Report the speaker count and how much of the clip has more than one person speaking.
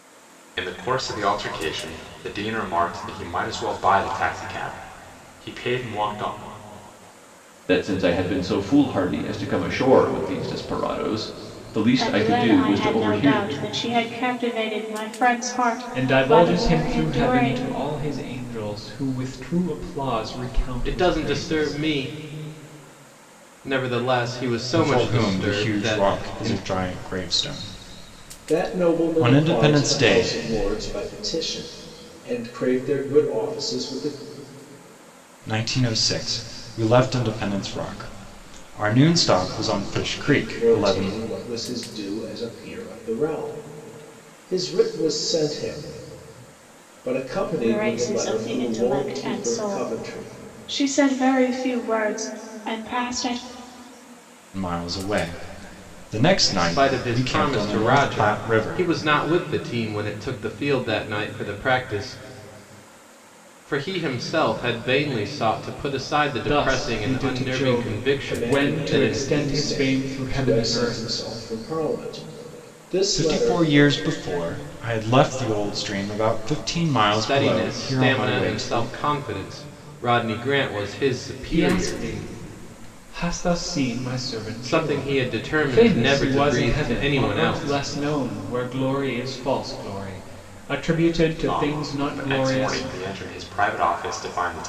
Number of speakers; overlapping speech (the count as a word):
seven, about 28%